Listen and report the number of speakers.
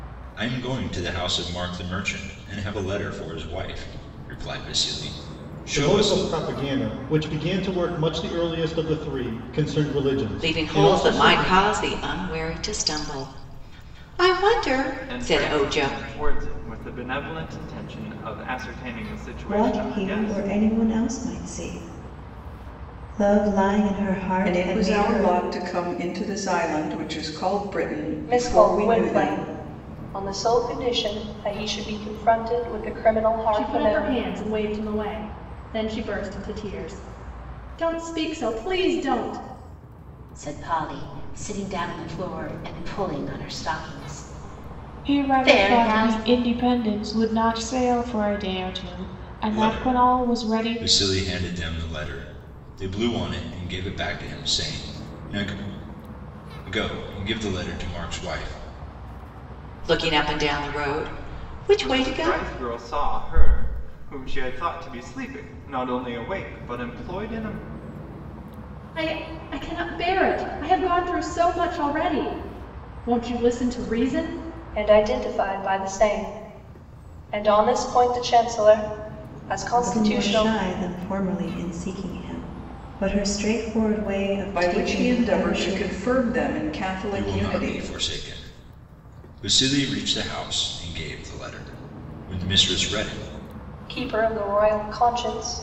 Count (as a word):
ten